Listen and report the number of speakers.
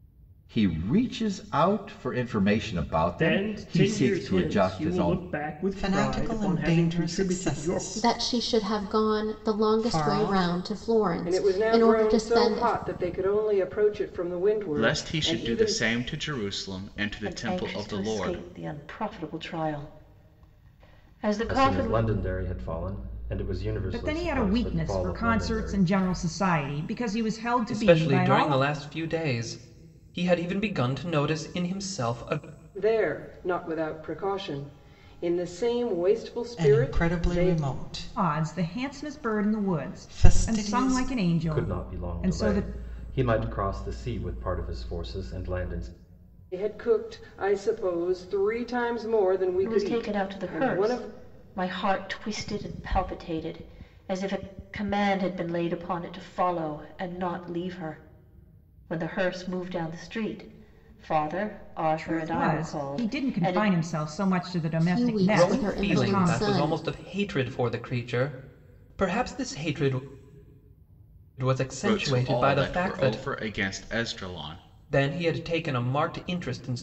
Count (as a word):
ten